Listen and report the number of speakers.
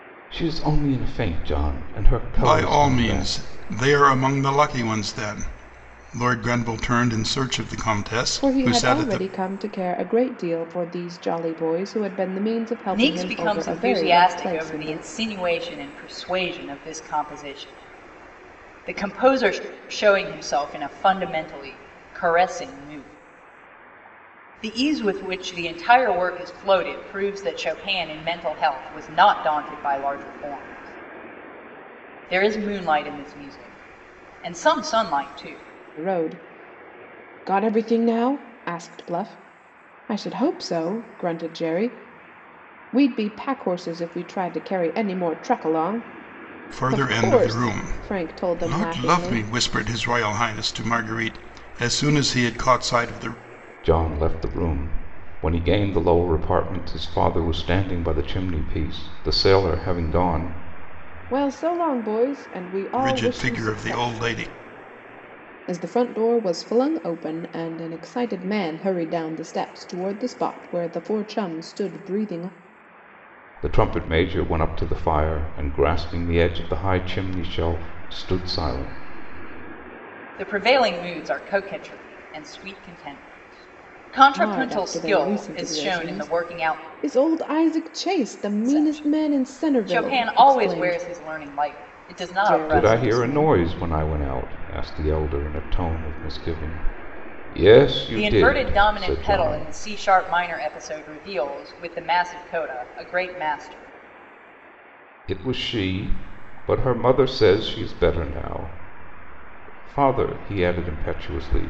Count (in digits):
4